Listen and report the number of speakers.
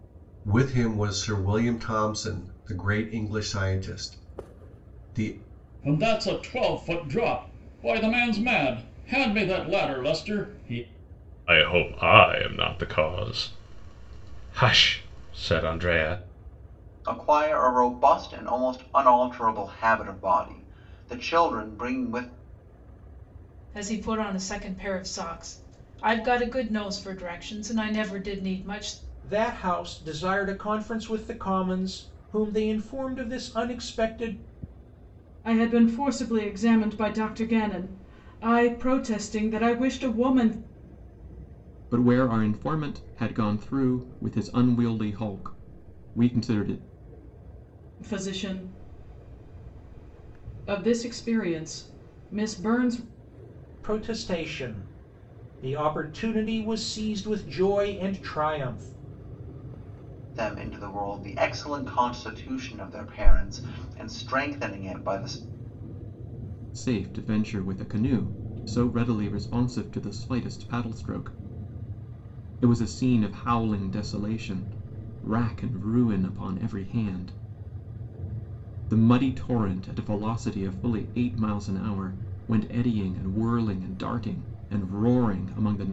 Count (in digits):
8